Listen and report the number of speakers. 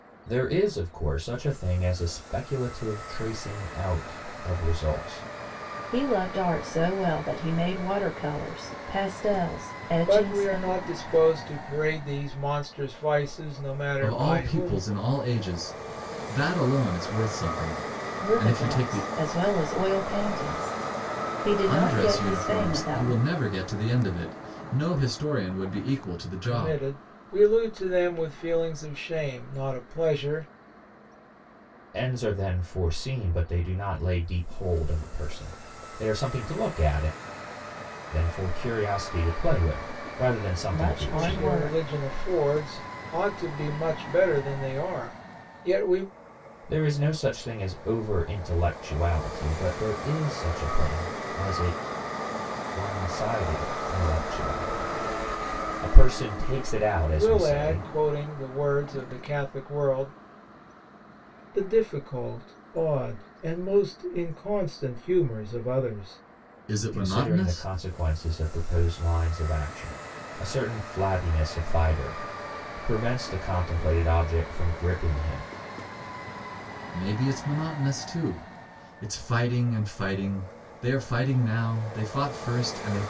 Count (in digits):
4